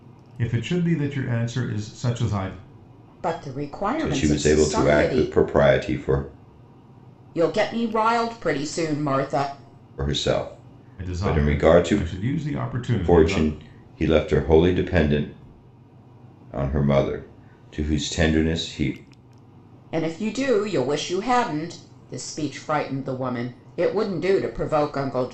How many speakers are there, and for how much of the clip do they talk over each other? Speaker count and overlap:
3, about 11%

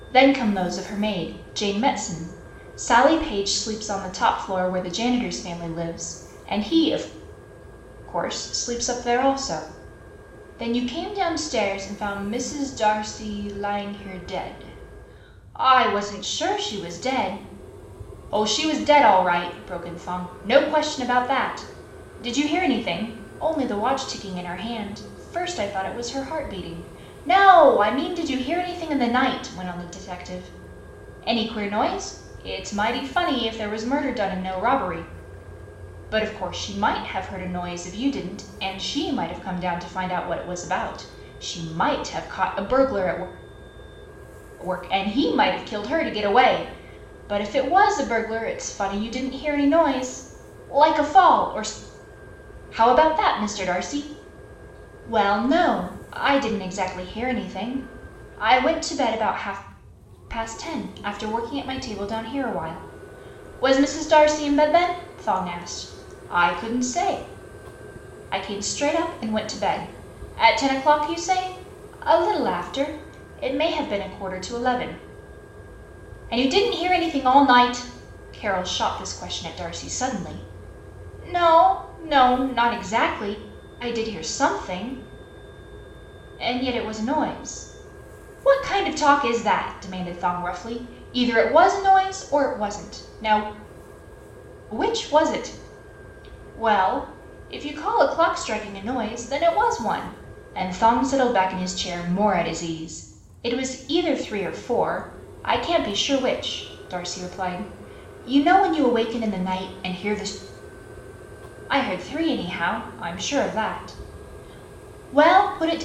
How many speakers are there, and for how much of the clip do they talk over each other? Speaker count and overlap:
1, no overlap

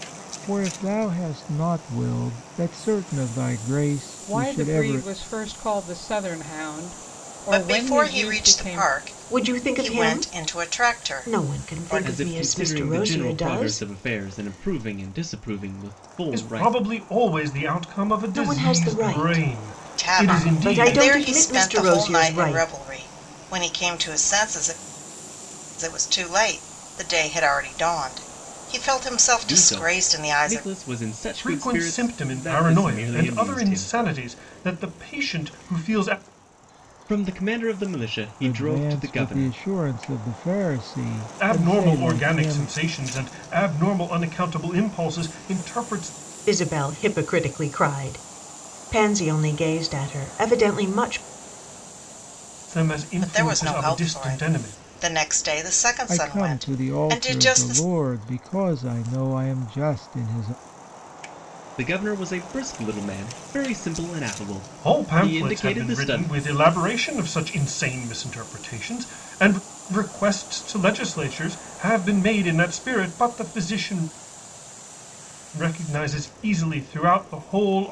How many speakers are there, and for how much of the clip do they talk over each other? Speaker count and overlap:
6, about 30%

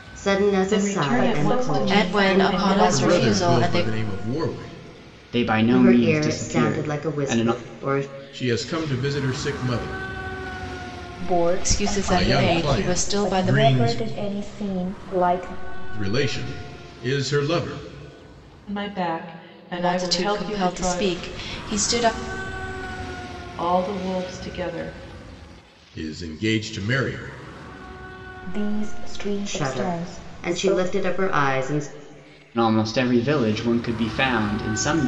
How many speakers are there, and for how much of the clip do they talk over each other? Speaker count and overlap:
6, about 30%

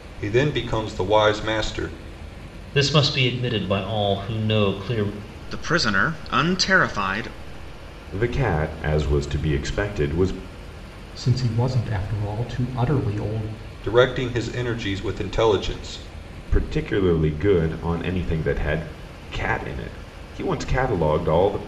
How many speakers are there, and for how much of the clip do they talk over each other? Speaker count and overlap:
5, no overlap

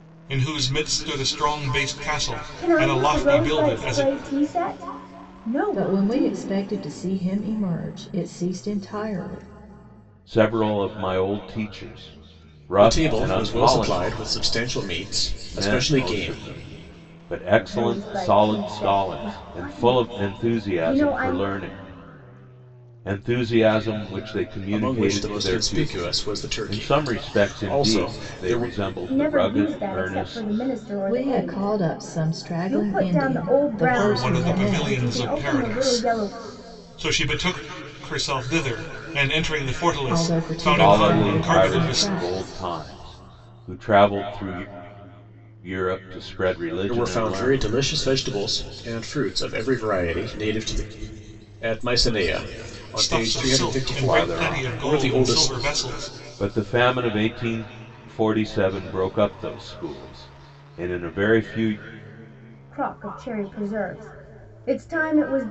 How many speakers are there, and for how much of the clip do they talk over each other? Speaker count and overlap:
5, about 38%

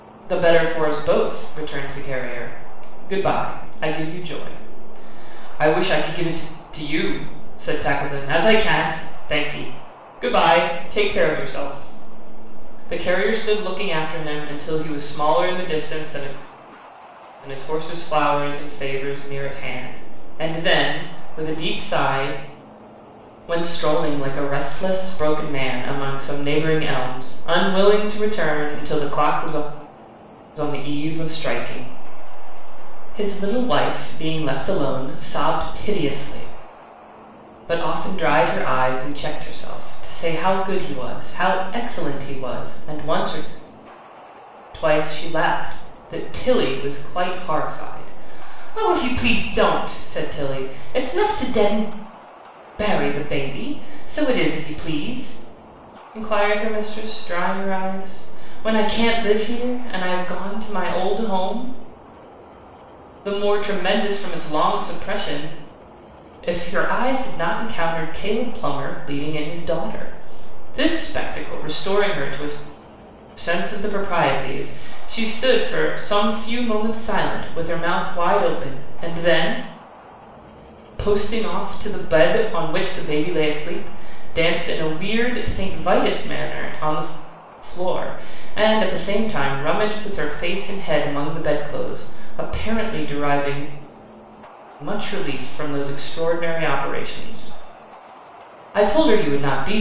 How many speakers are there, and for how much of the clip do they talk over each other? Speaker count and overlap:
1, no overlap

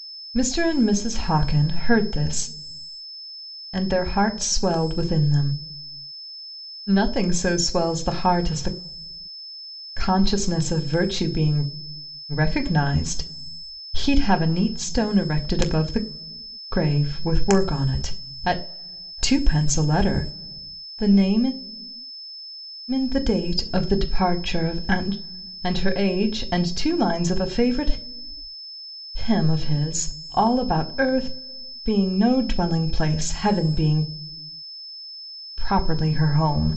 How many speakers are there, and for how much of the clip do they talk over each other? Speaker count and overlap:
1, no overlap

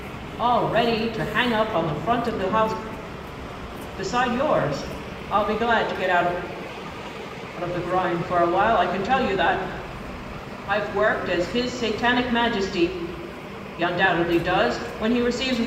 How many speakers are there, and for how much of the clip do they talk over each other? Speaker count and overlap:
1, no overlap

